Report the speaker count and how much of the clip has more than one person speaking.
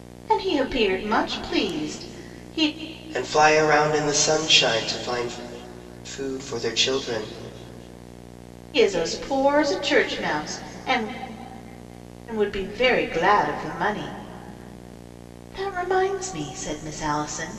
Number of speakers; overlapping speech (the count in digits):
2, no overlap